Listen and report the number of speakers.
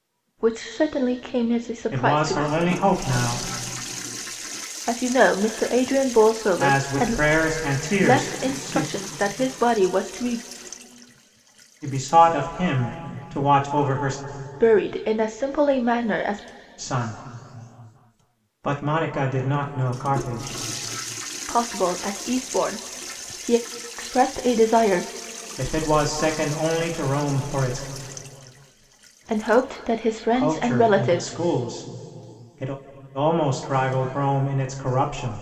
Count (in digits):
2